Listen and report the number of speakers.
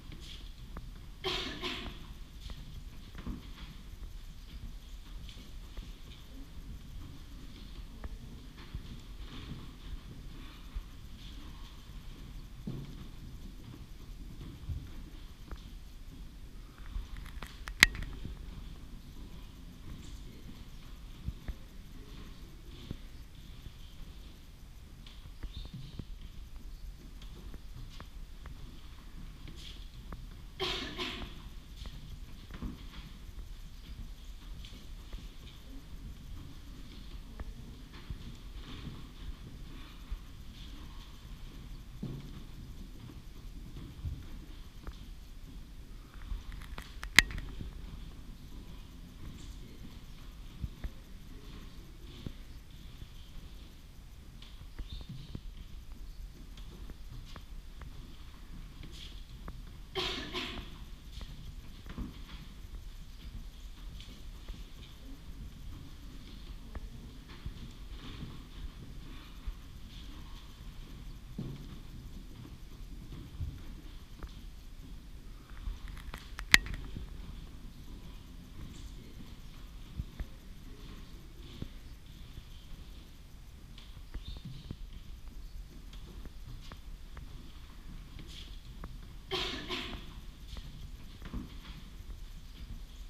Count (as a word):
zero